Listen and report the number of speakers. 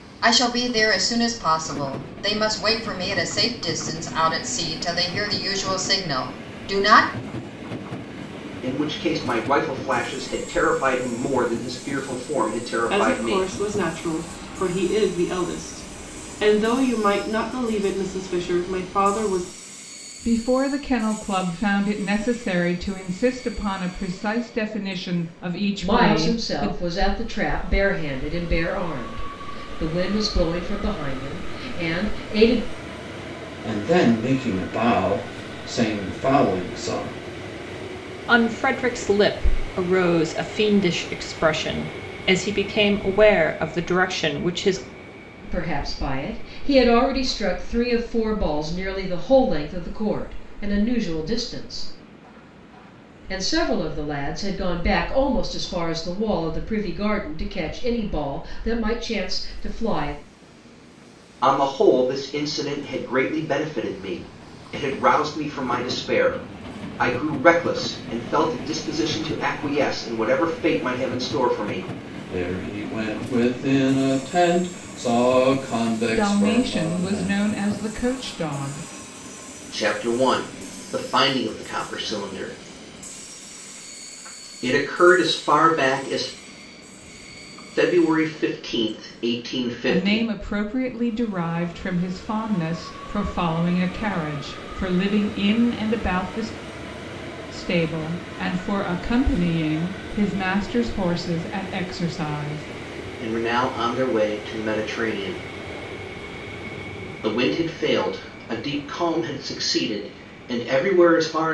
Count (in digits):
7